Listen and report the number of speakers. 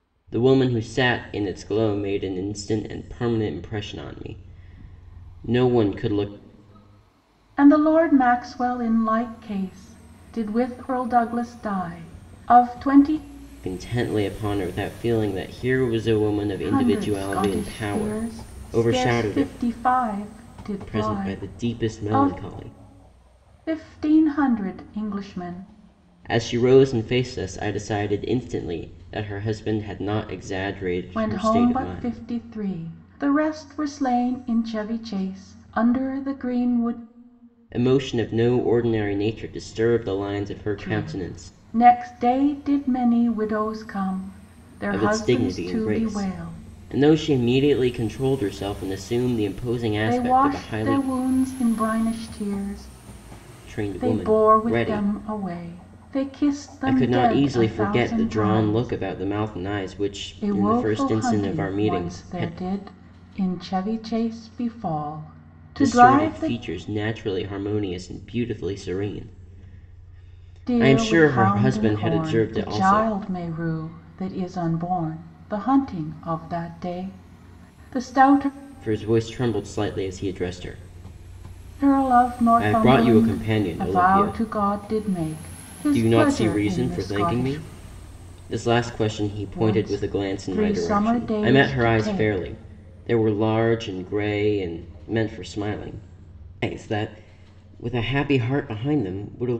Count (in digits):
2